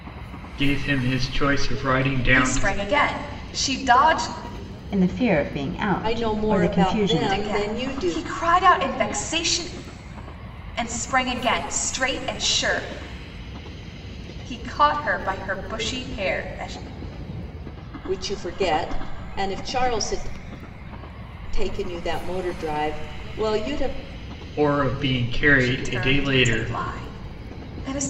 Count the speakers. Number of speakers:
four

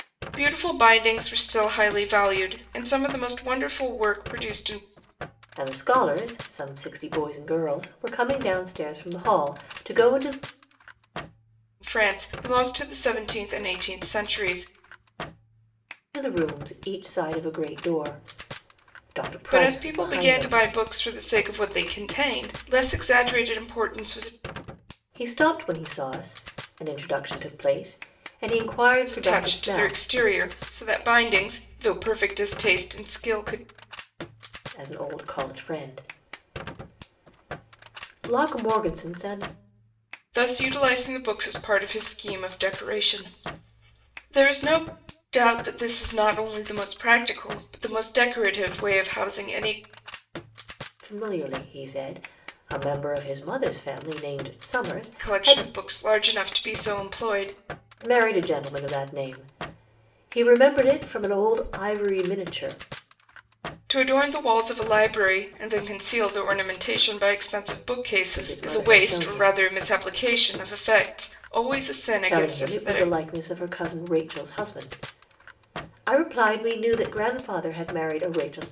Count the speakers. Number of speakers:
two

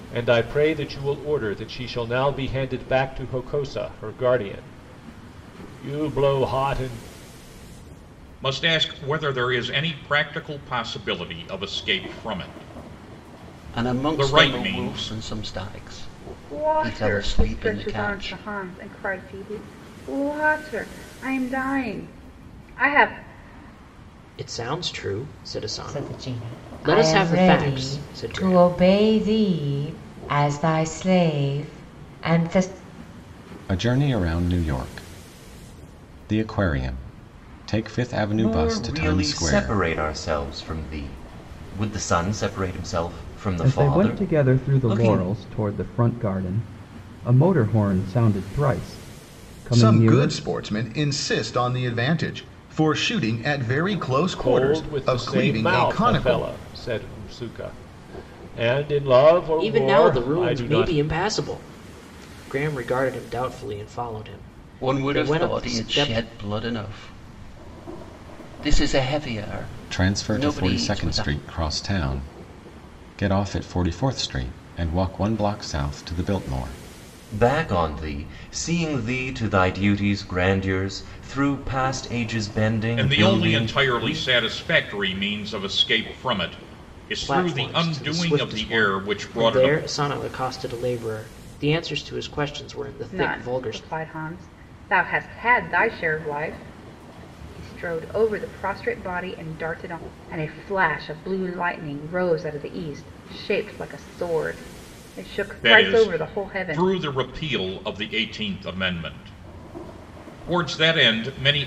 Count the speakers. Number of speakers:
ten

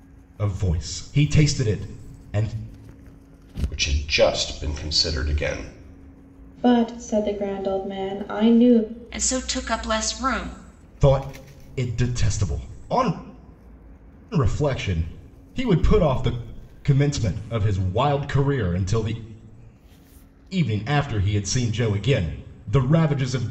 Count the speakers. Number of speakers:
four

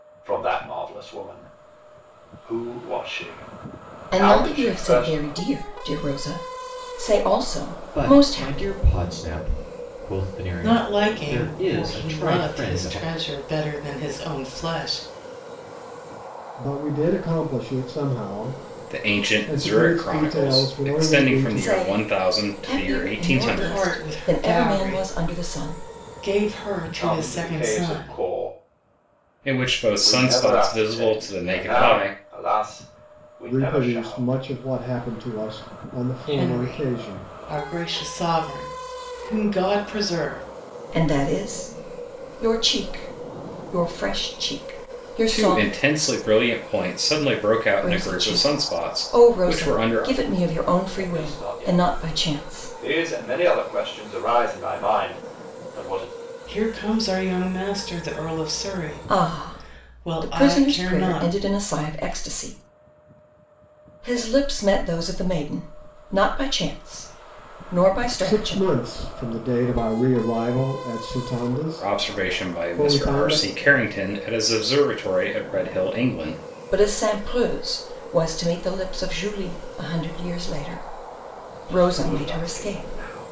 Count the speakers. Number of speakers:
six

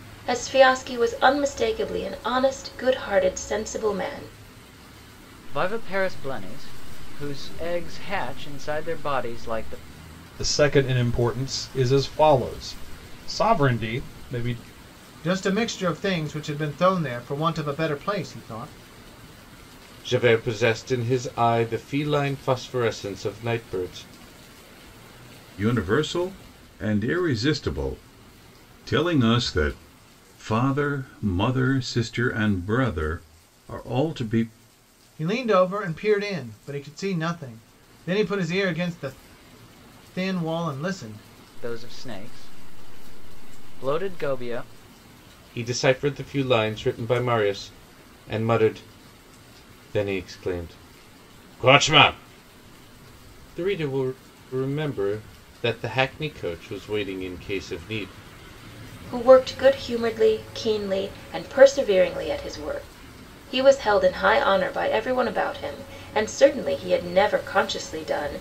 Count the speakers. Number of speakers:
six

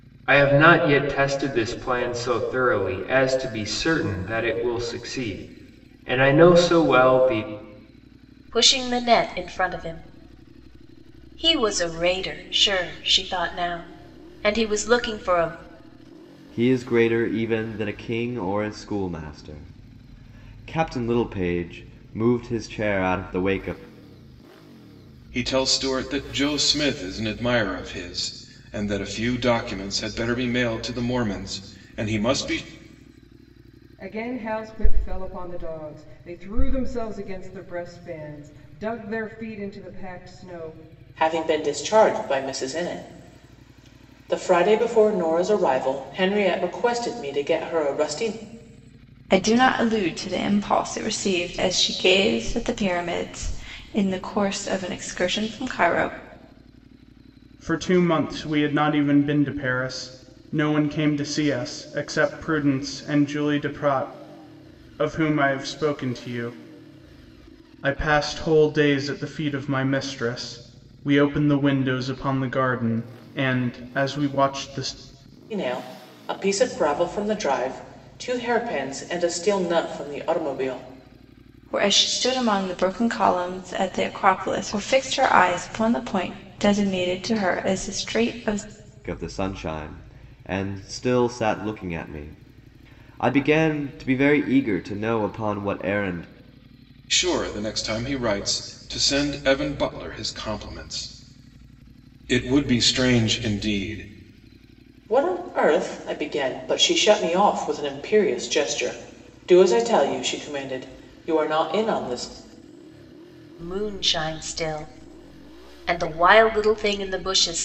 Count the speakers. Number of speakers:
eight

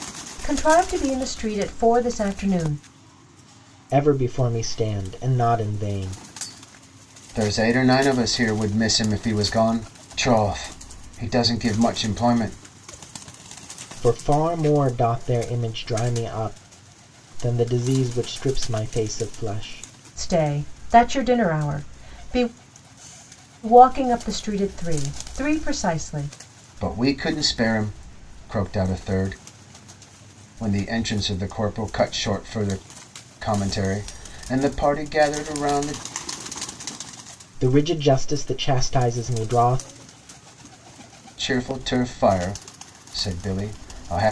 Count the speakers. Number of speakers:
three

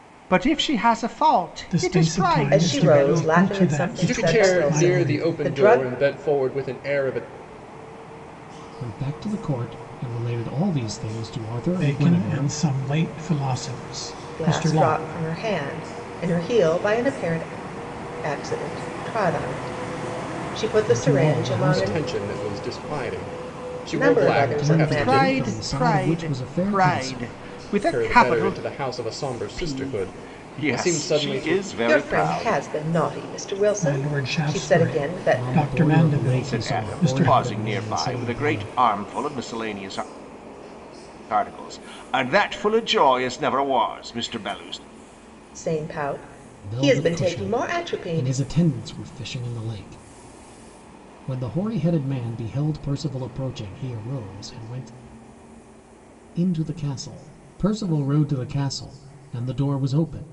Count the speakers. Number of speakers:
five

